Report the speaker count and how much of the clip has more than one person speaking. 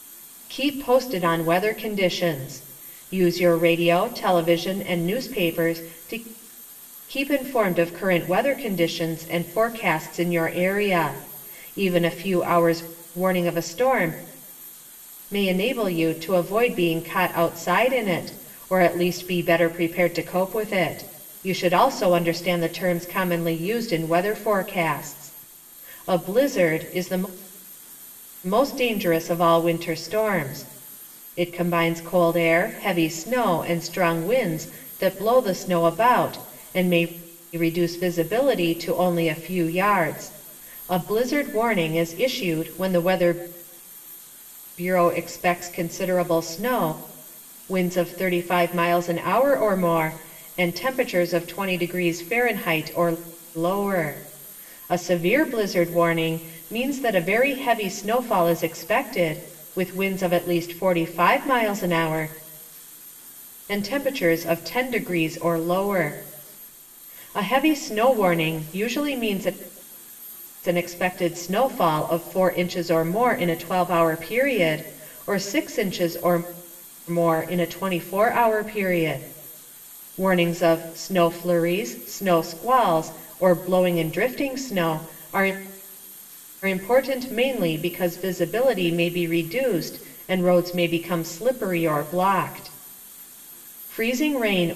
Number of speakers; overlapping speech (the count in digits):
1, no overlap